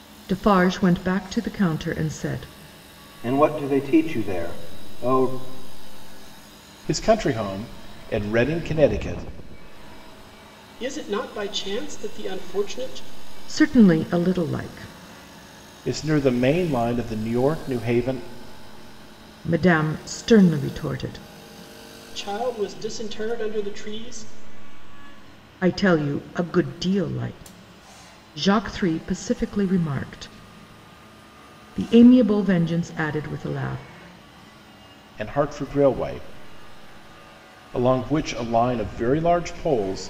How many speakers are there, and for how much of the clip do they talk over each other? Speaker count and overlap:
4, no overlap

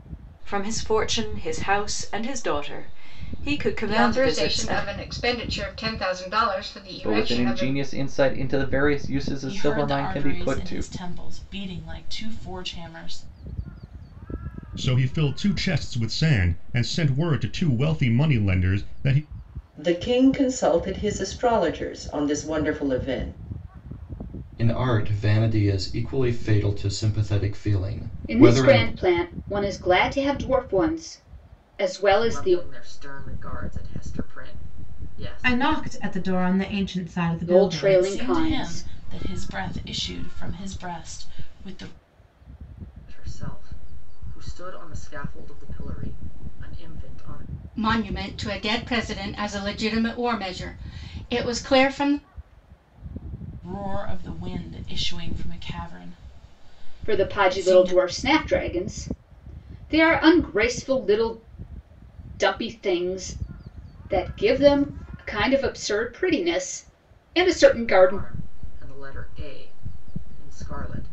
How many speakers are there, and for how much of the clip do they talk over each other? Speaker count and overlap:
10, about 12%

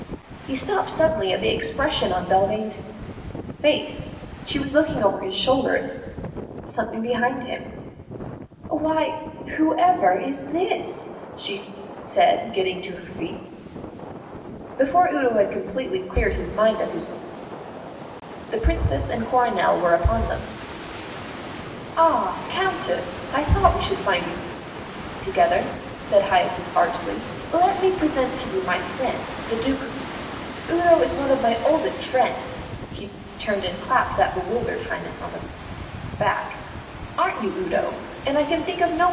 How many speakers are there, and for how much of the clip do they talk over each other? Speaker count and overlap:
1, no overlap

